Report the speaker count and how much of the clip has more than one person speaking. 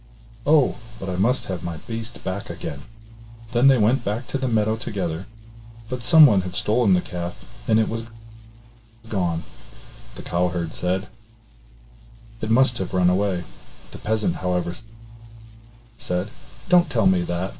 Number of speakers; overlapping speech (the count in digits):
1, no overlap